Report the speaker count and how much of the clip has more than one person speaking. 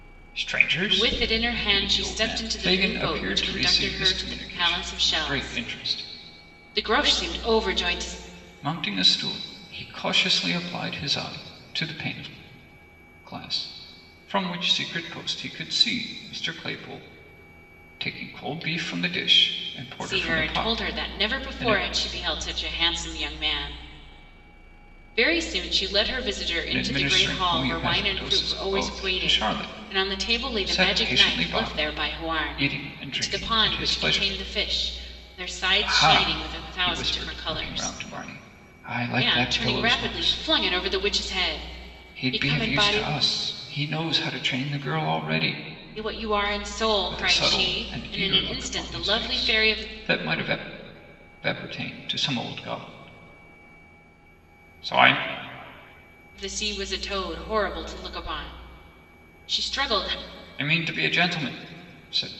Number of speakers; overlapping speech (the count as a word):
two, about 34%